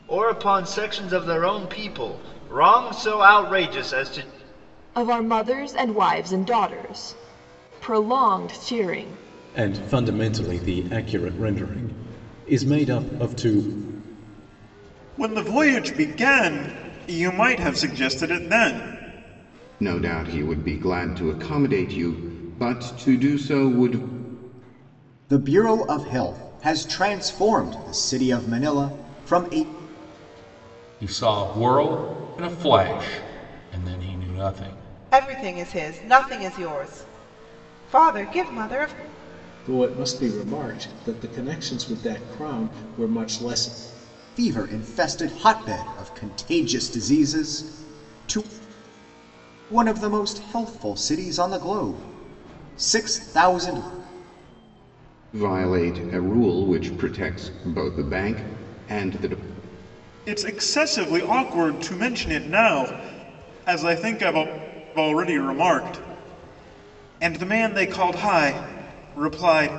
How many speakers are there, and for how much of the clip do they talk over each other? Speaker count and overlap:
nine, no overlap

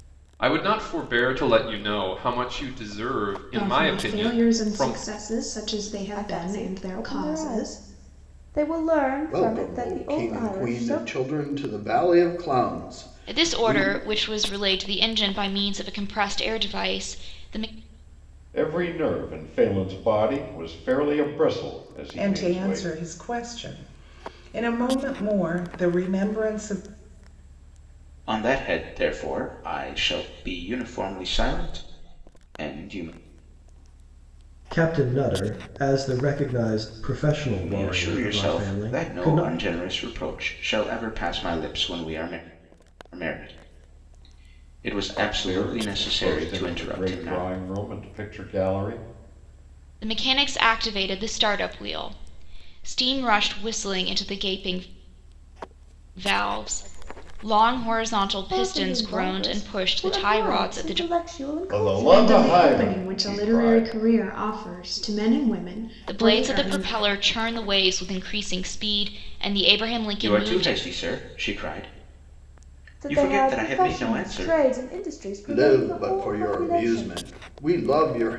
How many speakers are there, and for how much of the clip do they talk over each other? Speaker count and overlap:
nine, about 26%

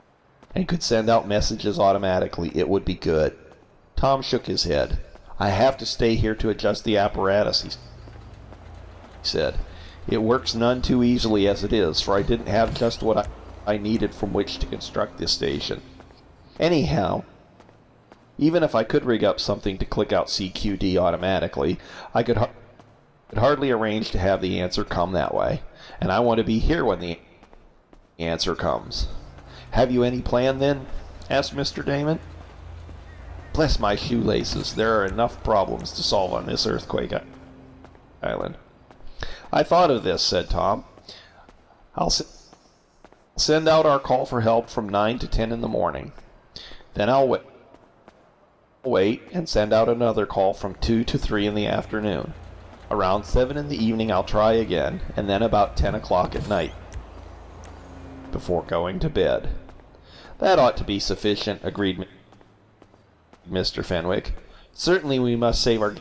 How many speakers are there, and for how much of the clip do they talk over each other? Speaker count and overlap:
one, no overlap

